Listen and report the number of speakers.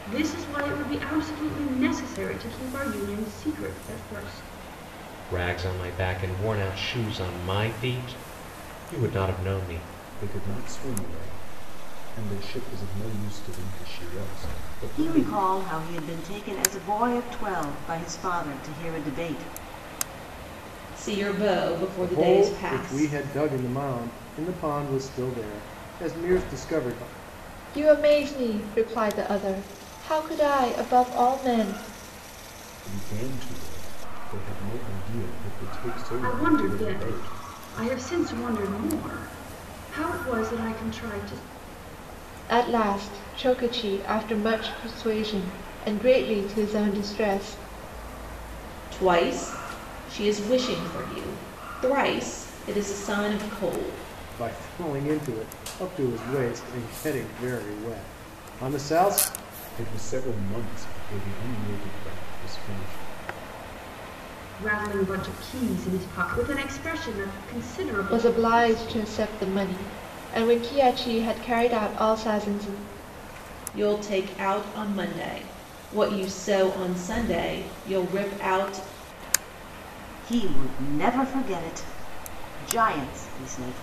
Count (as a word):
seven